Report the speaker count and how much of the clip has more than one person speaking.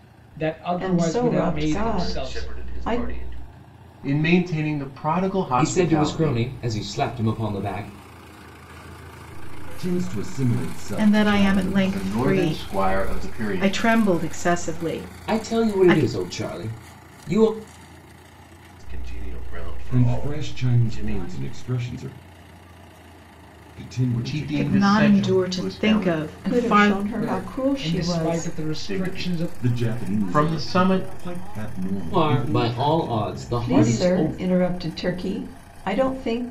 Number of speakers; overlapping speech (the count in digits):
8, about 59%